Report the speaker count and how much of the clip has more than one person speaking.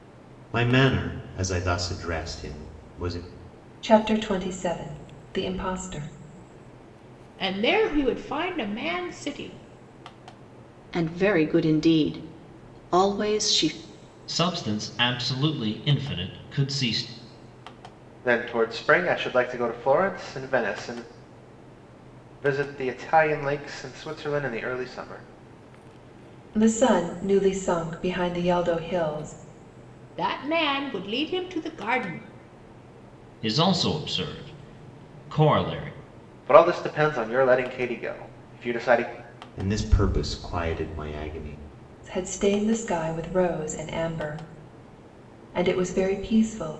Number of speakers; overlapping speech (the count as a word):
six, no overlap